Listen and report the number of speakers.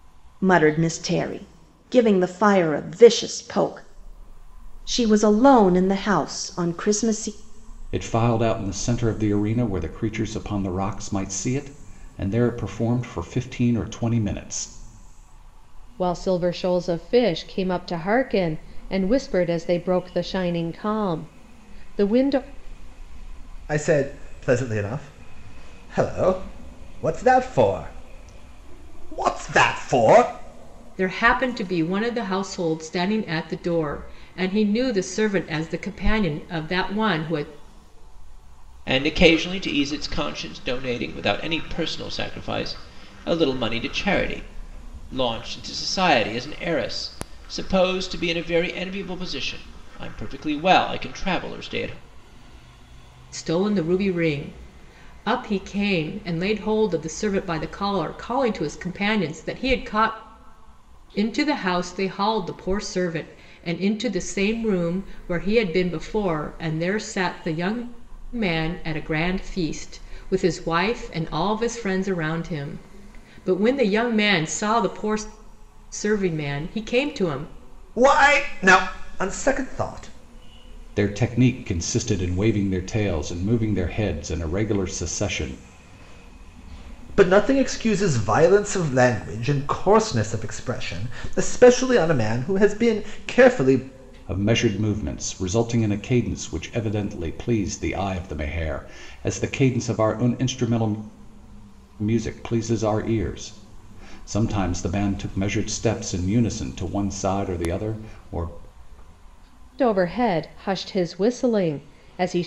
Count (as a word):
six